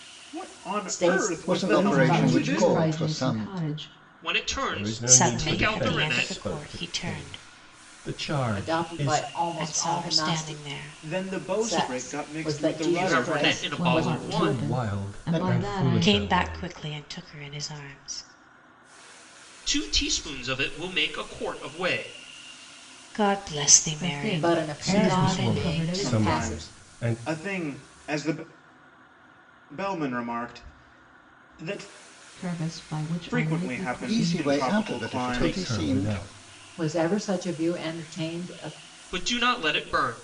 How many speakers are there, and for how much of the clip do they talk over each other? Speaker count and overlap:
seven, about 48%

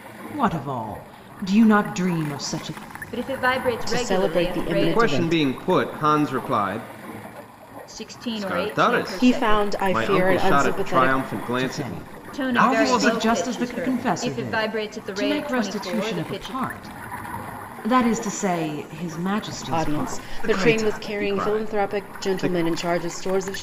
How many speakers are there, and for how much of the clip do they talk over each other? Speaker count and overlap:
four, about 50%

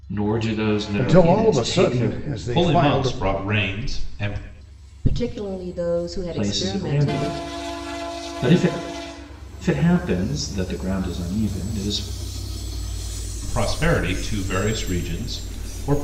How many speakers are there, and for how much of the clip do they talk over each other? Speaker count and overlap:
four, about 20%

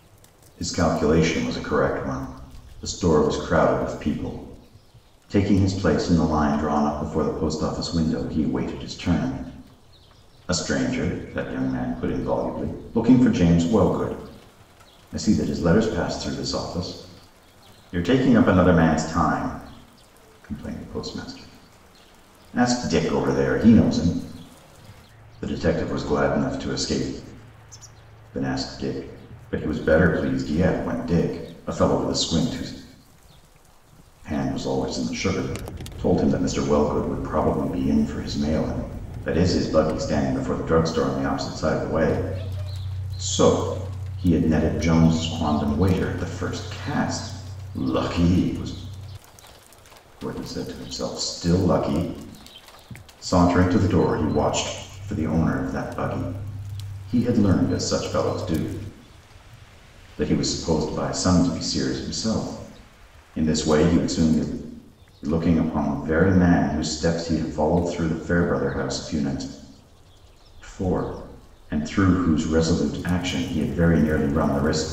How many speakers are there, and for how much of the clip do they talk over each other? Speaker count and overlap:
one, no overlap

